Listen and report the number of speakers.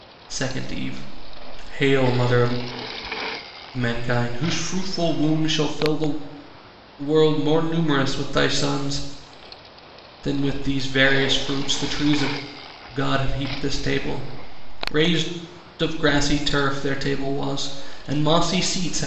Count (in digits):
1